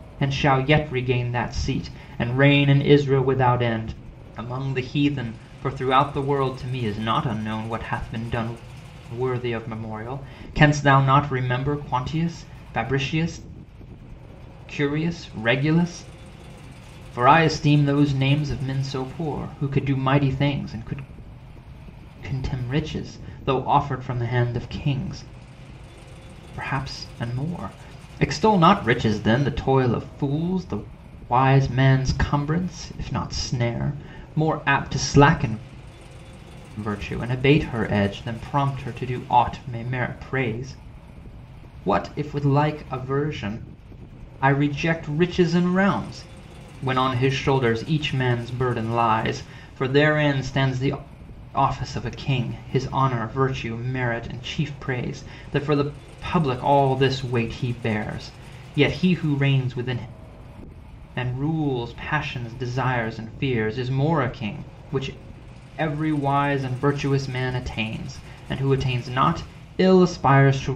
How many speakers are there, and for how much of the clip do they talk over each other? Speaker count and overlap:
one, no overlap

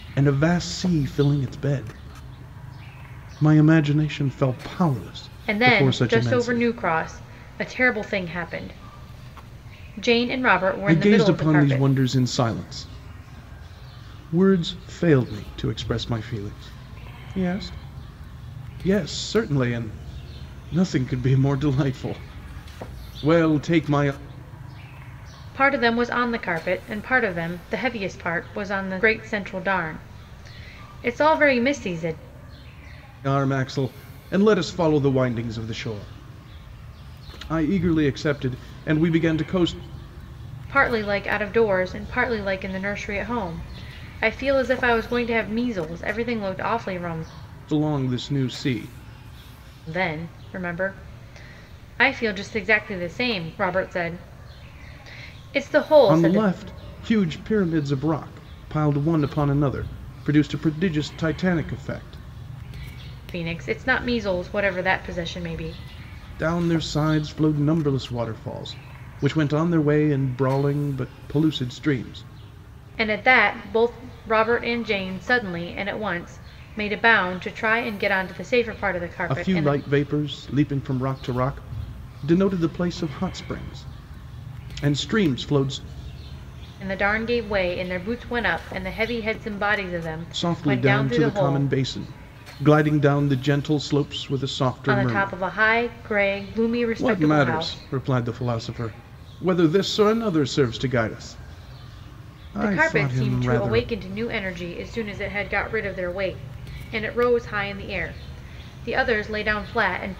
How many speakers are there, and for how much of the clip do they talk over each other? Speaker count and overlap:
two, about 7%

